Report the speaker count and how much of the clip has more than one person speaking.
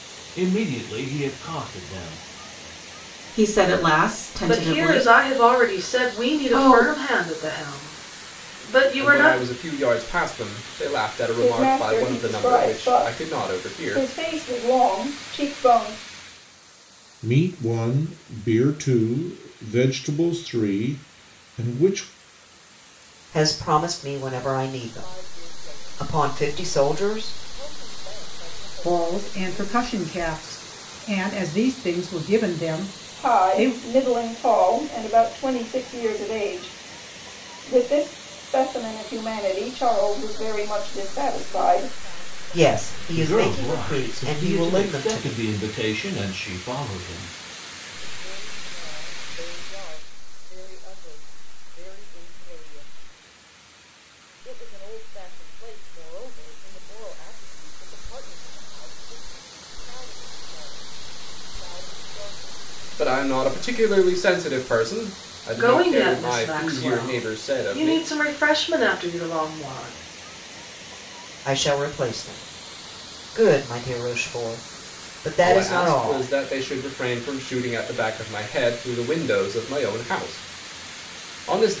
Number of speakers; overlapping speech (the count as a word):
nine, about 24%